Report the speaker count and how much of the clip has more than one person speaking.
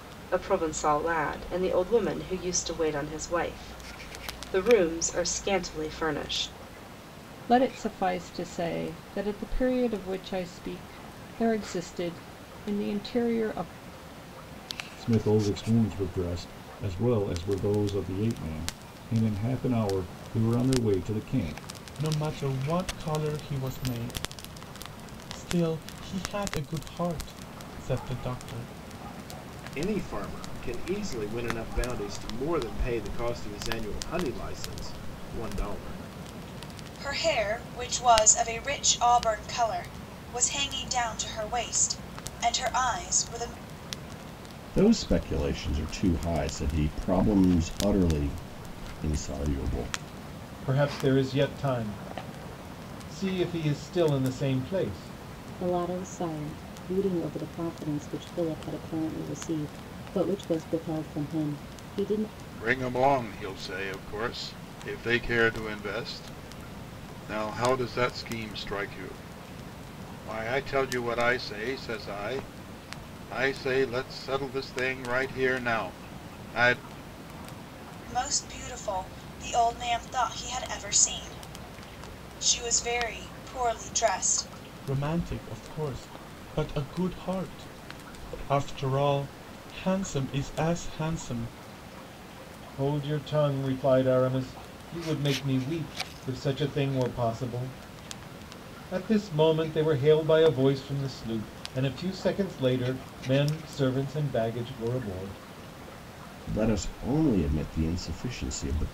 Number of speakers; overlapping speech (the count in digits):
10, no overlap